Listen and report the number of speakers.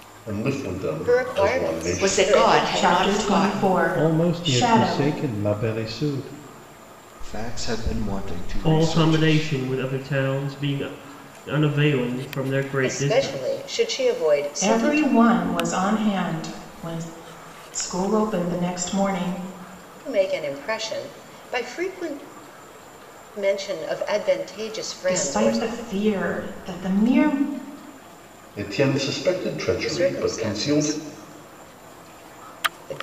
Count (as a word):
seven